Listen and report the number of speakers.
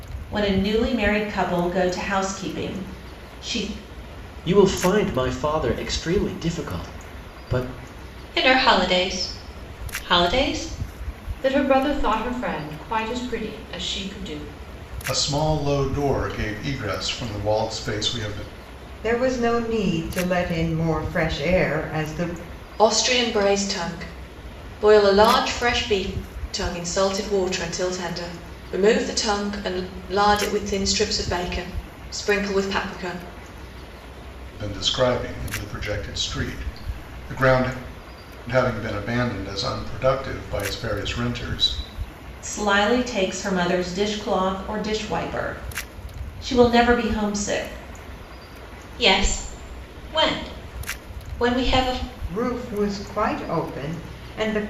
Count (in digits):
7